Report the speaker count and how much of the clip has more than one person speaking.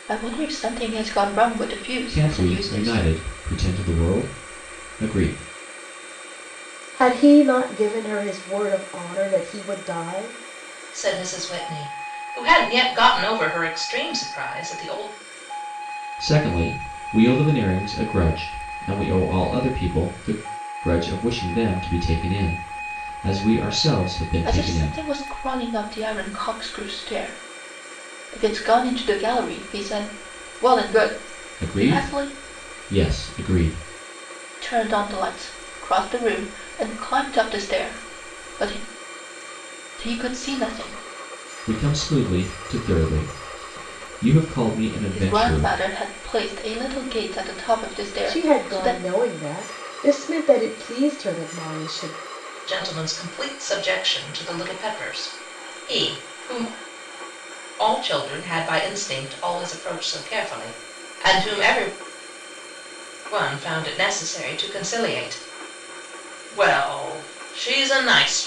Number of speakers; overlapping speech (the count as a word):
four, about 6%